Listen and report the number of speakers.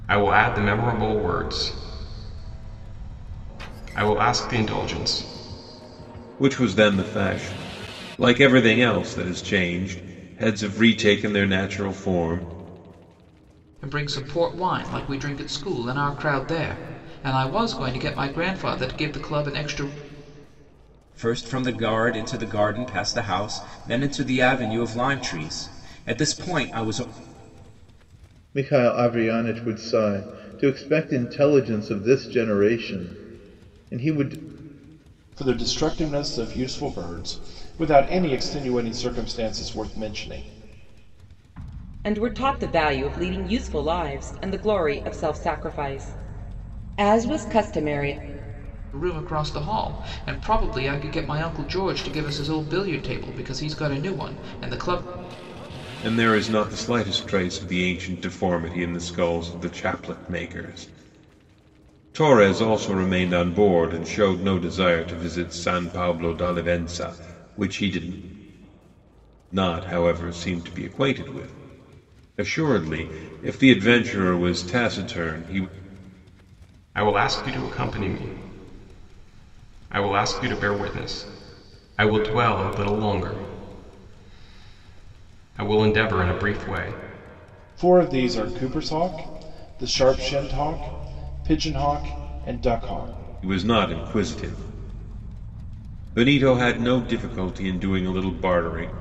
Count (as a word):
seven